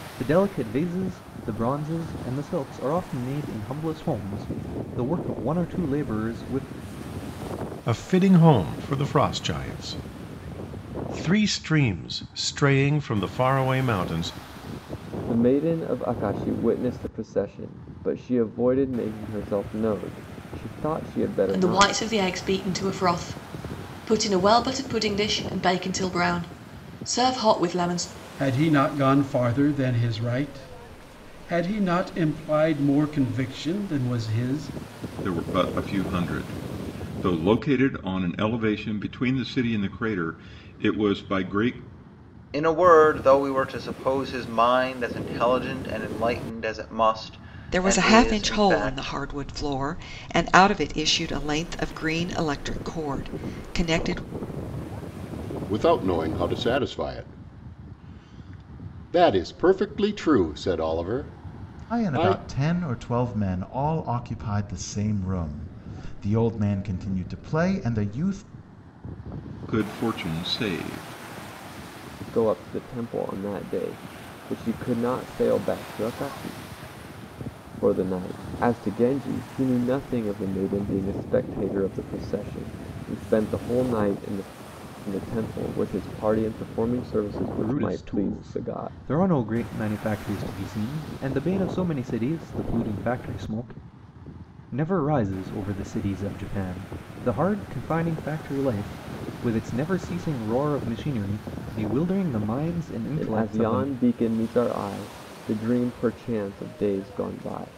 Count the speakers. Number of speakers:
10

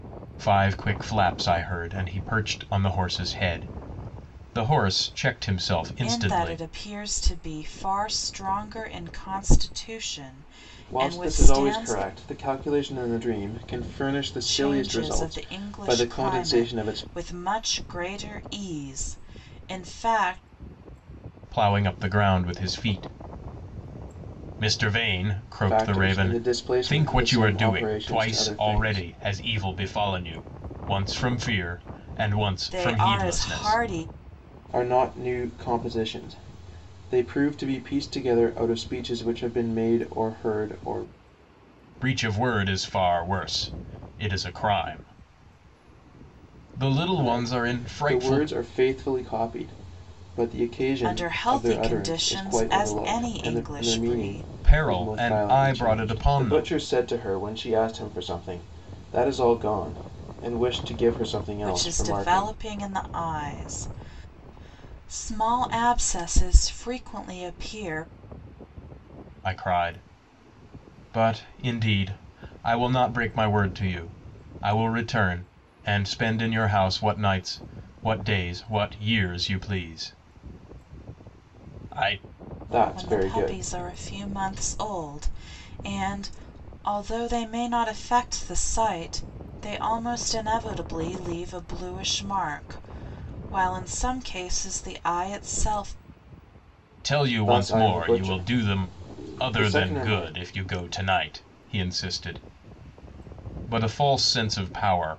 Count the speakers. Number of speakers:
3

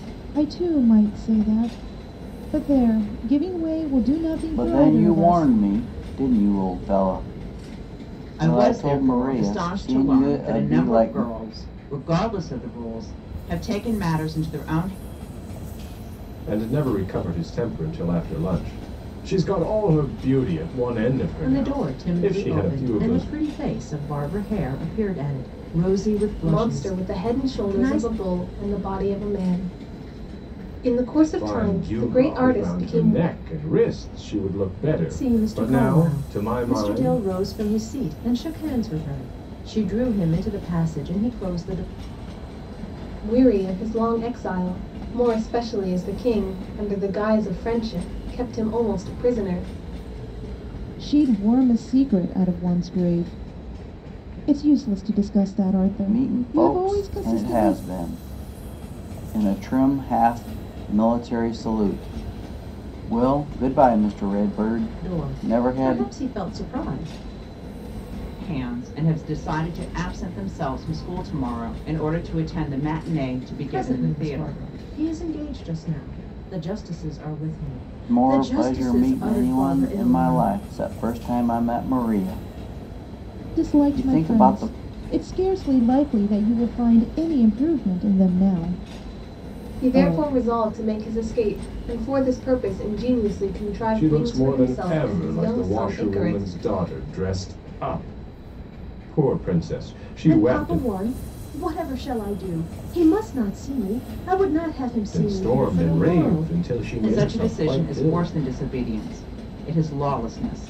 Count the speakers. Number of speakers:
6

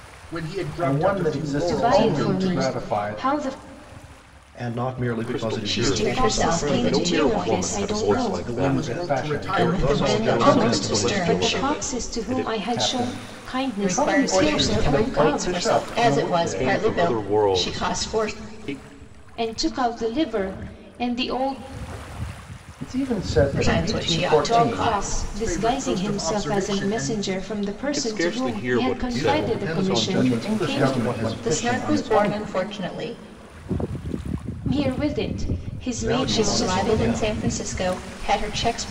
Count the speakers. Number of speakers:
6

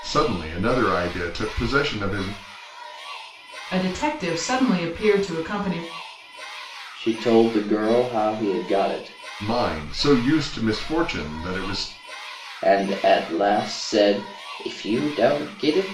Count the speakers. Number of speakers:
3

